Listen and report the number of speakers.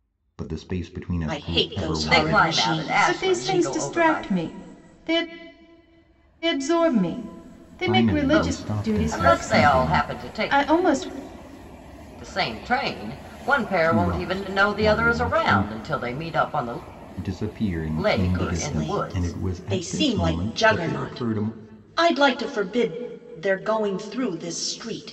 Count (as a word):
four